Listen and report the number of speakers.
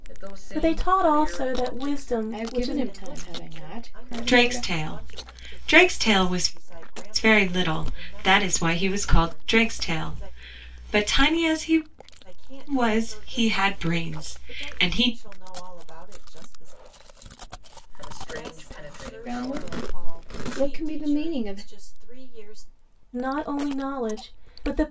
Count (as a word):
five